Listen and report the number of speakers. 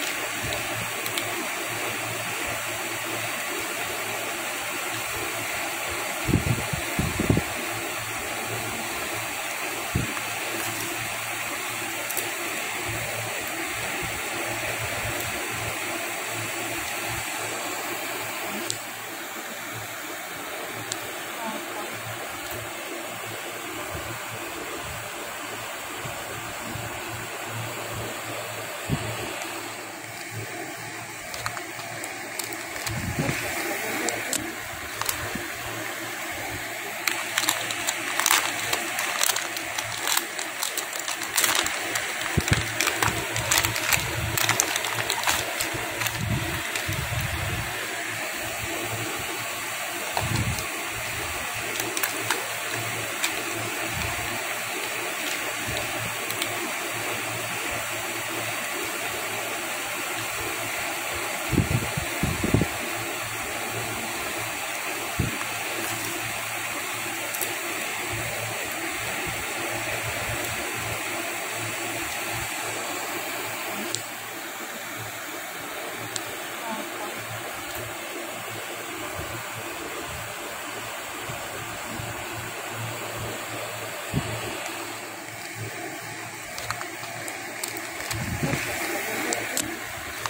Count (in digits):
0